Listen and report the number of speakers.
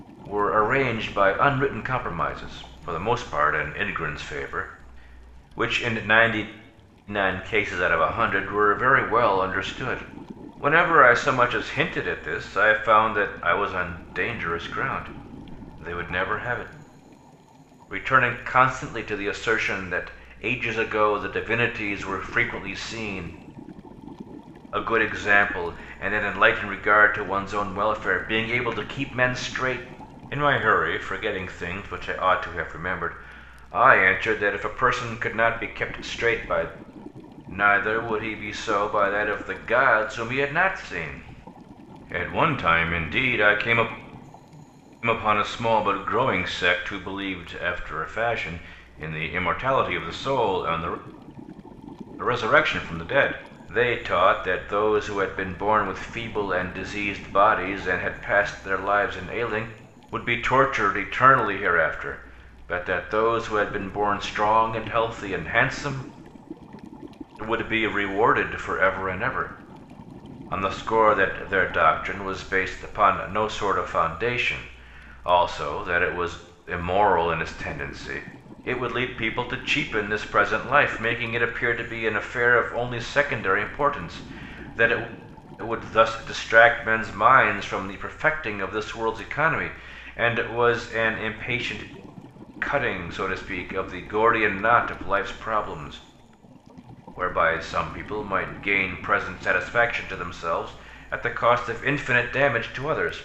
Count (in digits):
1